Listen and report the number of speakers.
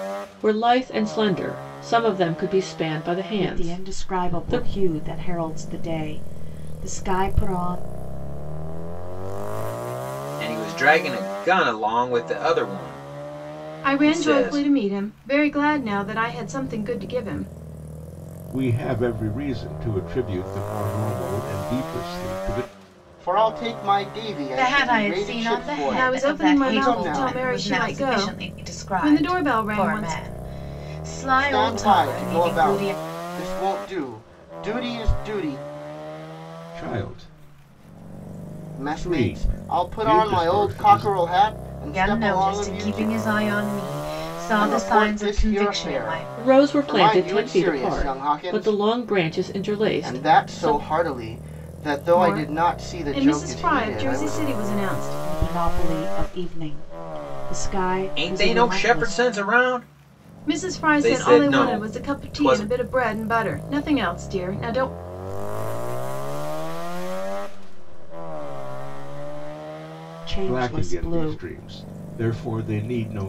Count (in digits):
8